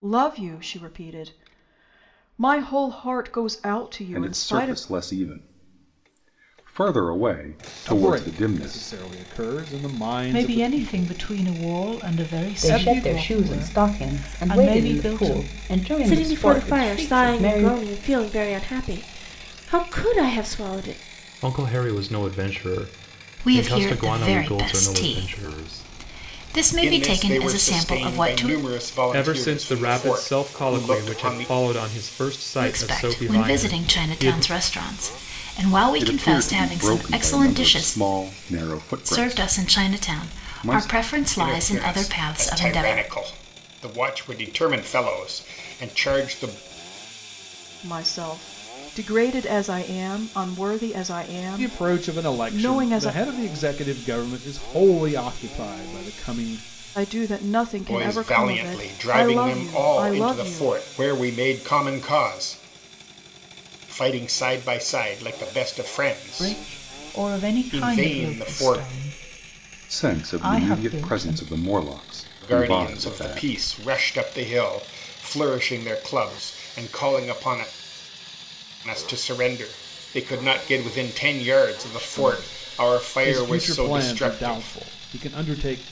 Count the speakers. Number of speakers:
ten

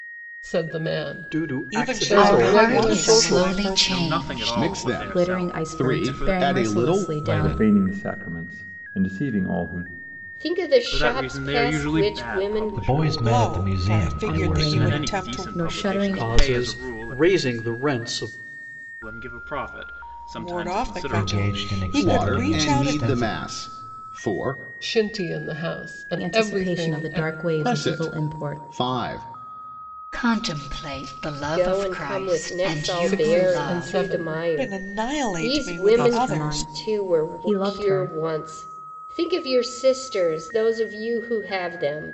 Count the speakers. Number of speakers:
ten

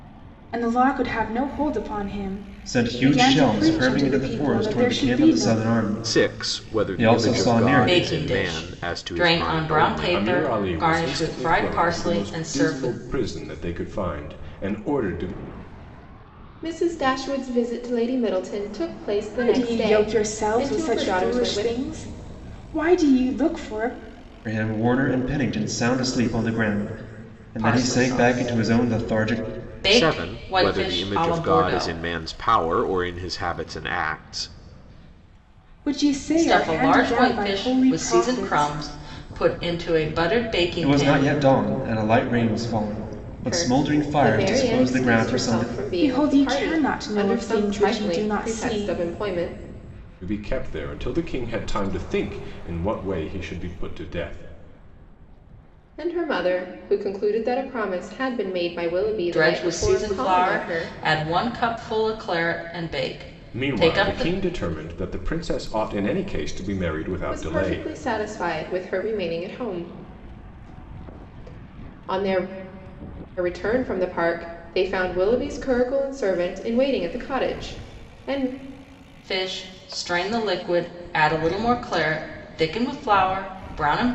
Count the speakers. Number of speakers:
six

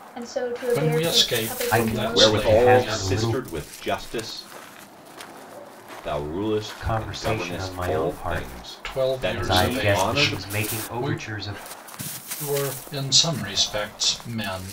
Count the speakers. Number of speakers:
four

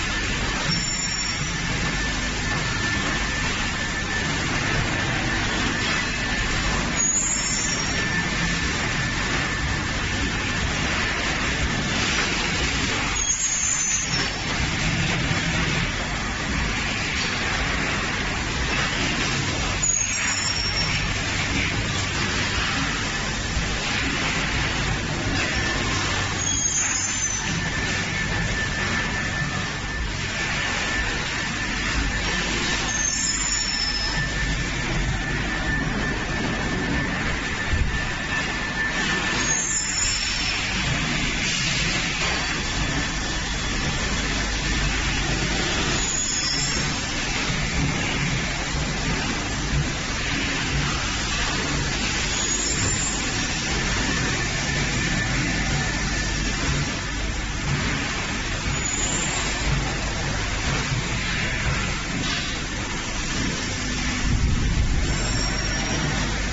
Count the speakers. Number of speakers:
zero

